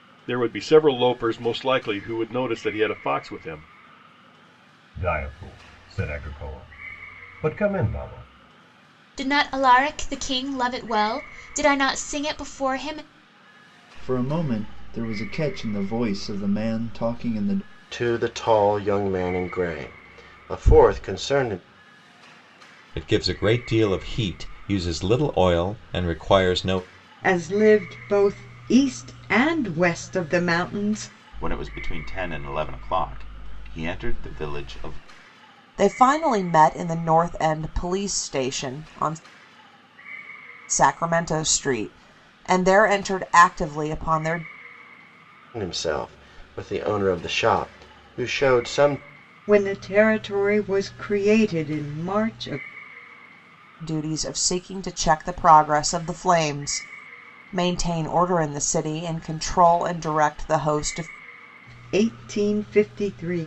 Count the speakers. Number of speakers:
nine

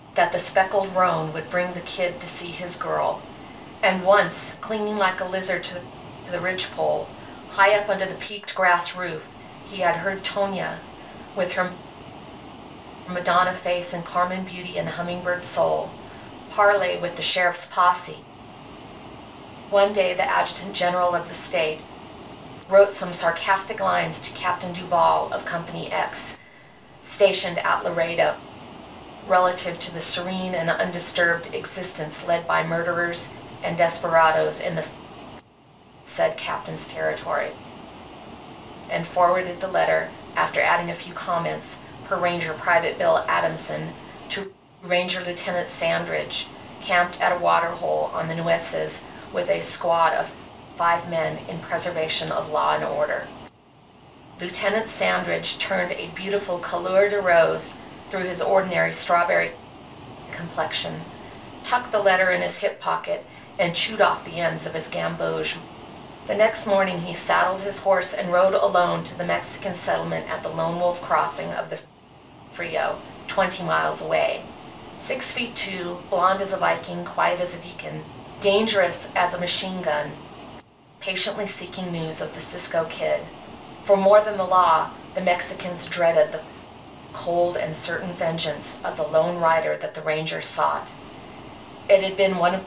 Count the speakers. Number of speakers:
one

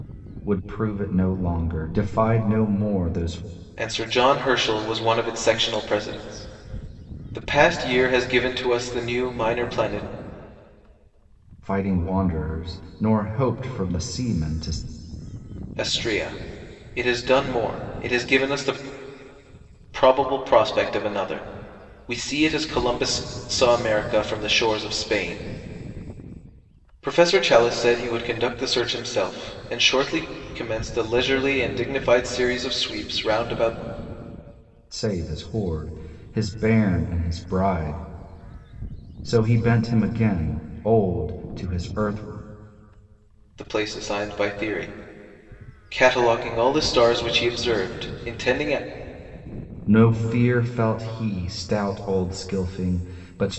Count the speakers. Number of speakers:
two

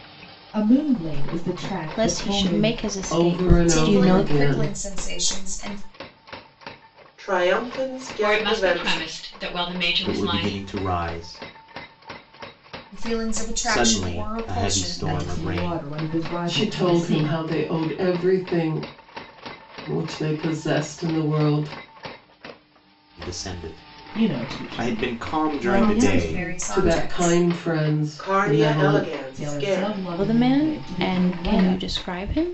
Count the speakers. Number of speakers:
seven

